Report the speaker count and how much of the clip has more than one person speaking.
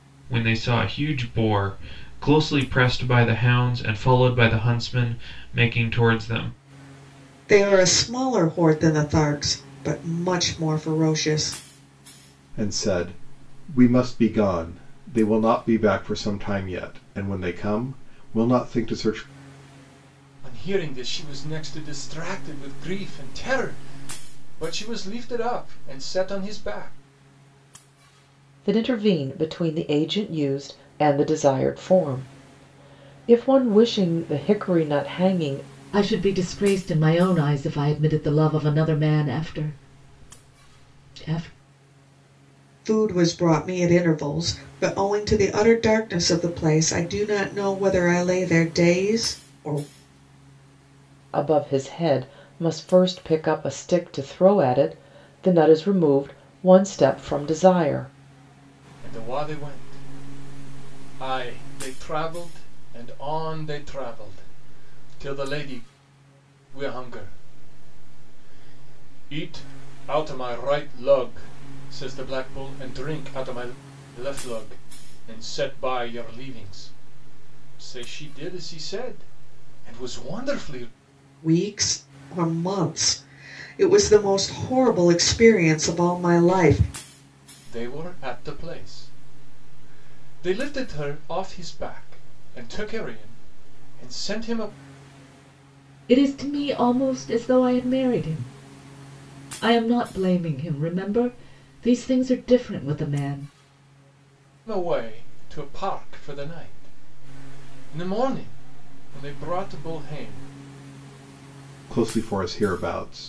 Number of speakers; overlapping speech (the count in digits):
6, no overlap